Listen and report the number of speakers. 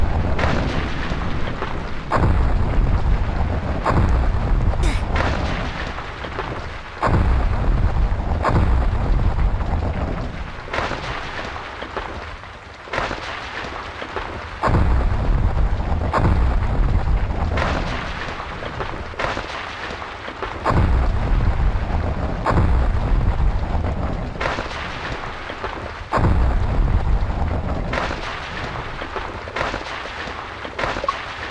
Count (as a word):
zero